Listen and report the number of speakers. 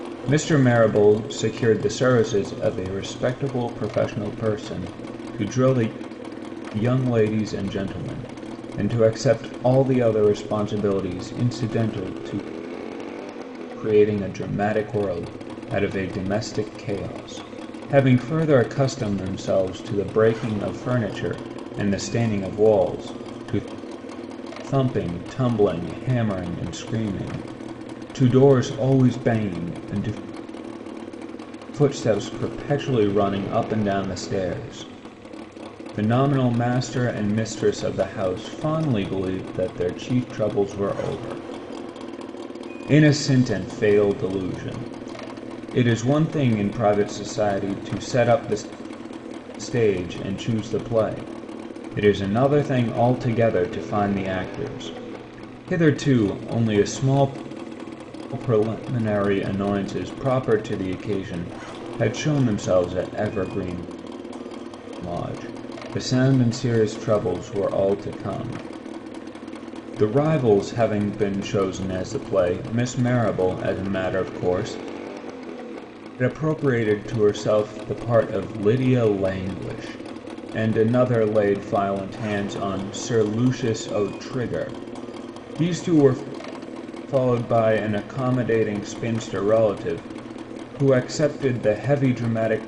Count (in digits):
1